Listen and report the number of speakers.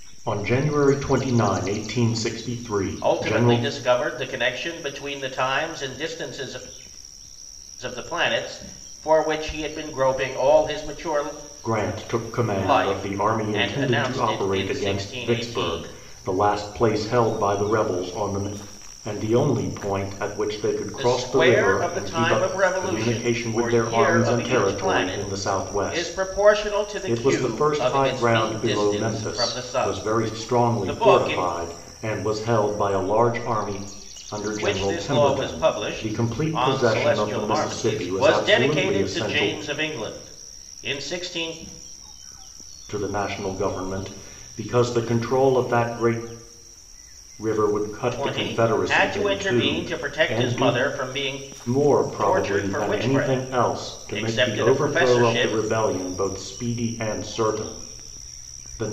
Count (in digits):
2